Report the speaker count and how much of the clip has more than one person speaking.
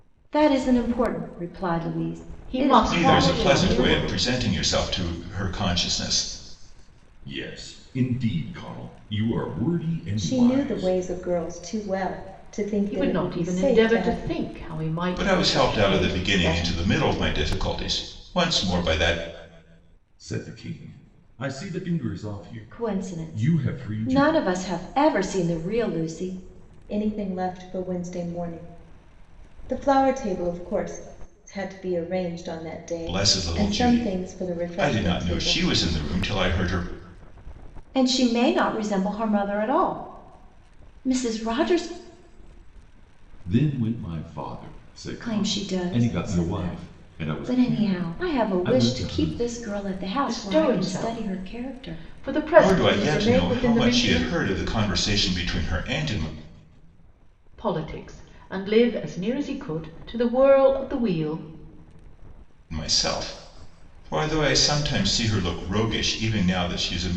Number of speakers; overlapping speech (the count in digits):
5, about 27%